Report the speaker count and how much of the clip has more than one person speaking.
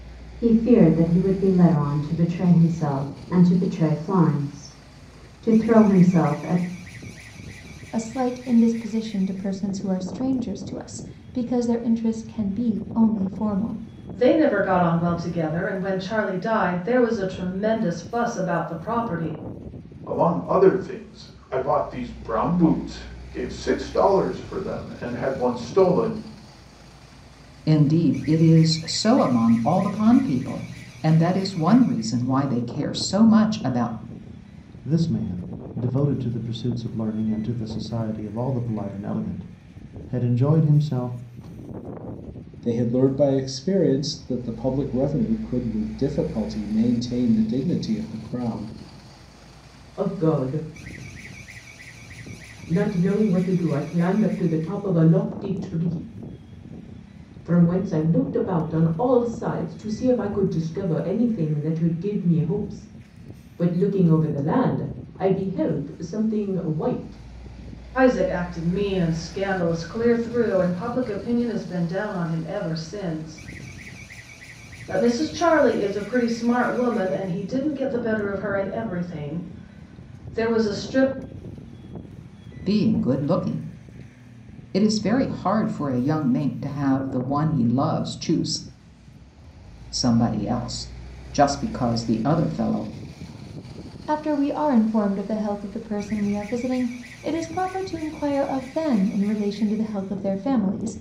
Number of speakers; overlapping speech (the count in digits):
8, no overlap